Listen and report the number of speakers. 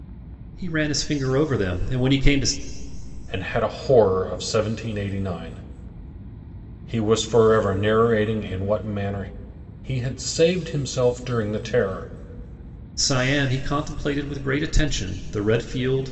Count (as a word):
two